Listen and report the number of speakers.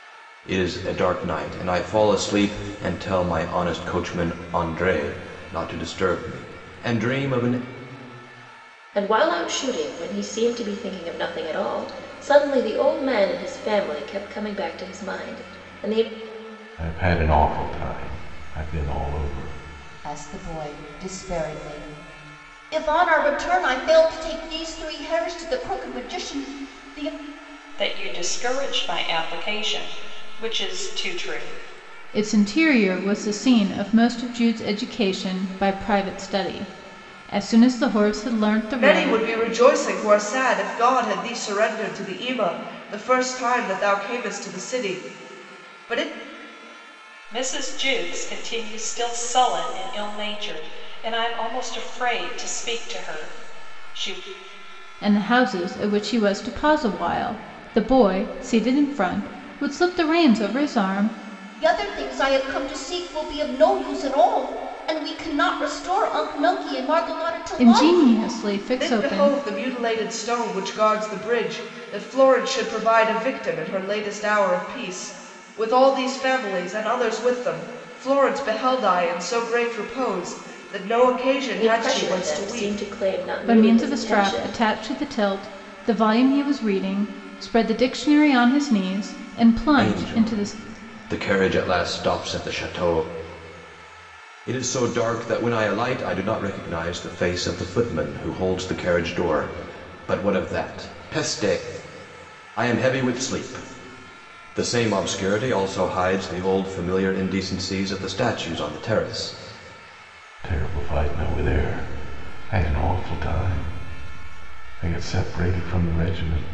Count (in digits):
7